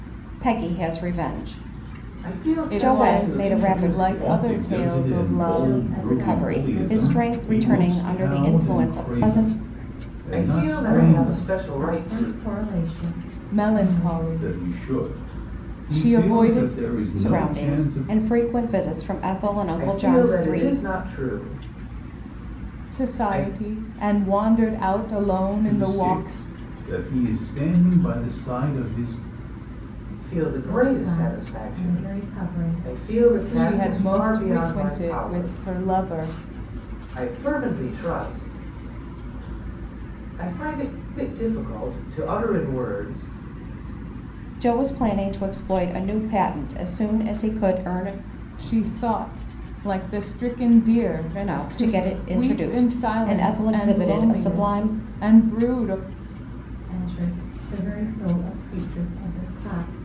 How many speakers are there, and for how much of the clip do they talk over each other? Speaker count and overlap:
5, about 39%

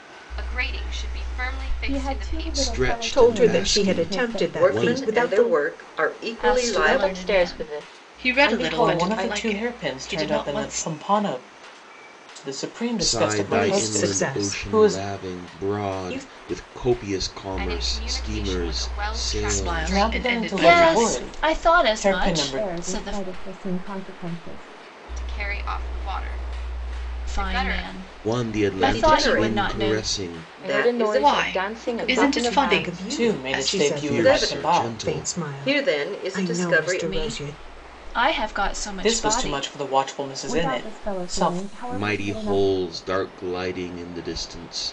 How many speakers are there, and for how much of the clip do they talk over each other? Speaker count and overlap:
9, about 65%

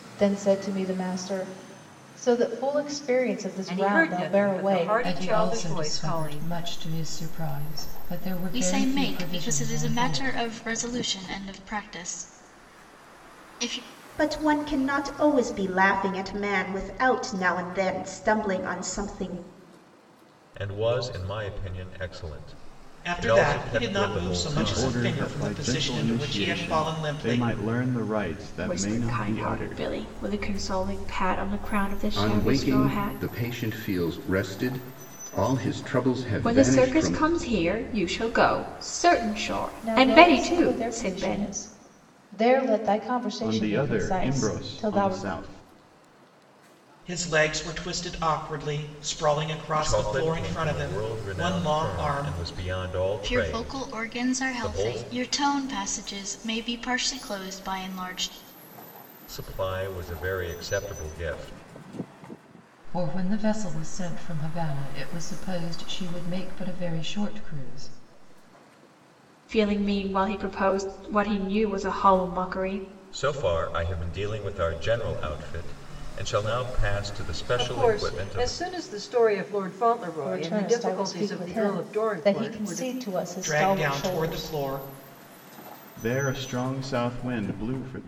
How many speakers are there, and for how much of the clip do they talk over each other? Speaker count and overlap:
10, about 29%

